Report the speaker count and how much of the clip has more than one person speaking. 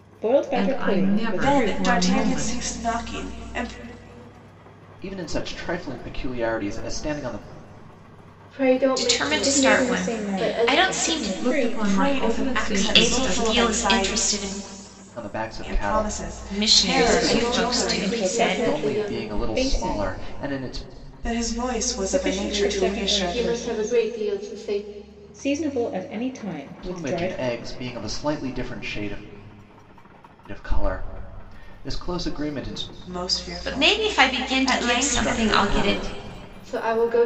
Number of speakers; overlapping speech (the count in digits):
6, about 46%